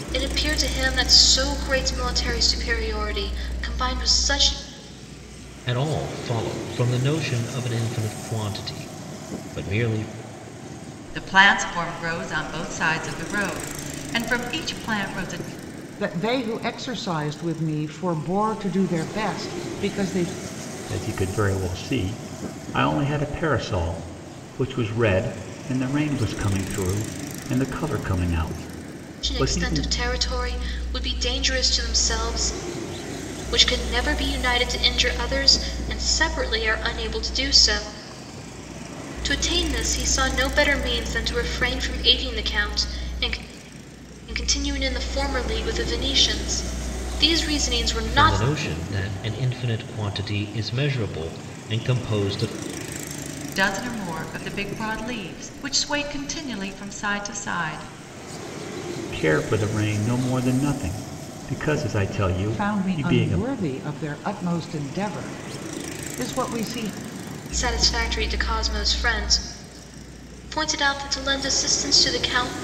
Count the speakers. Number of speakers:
five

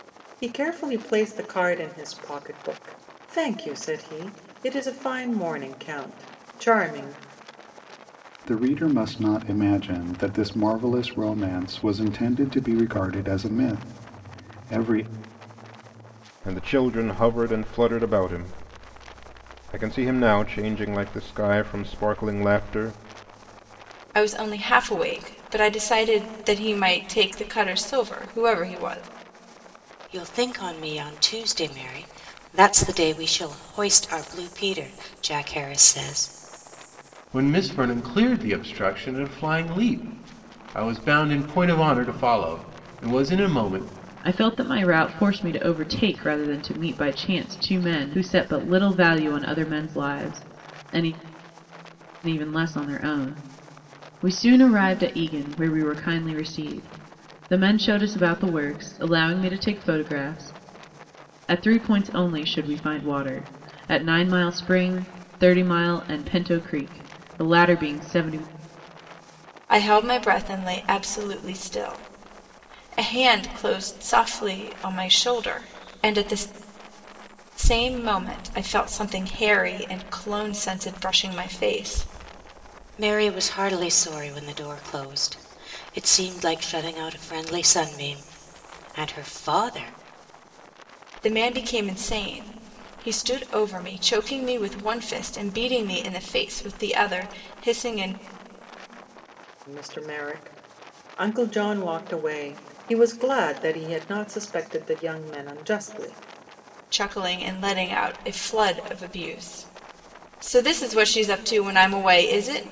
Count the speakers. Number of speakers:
seven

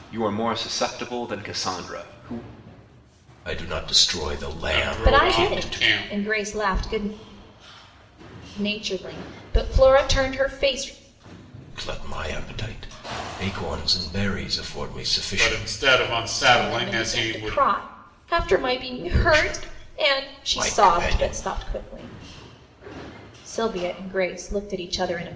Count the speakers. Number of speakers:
four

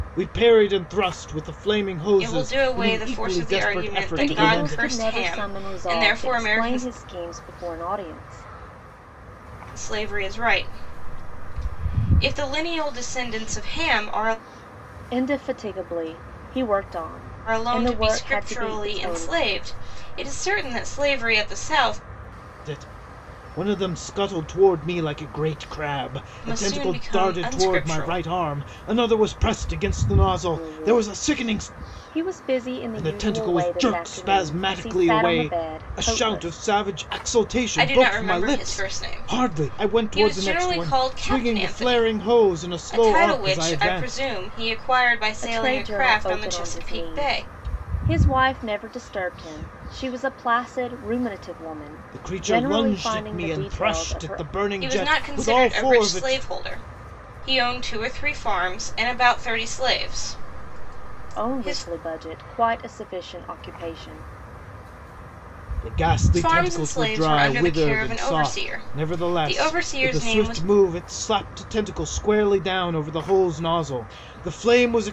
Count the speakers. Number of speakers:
three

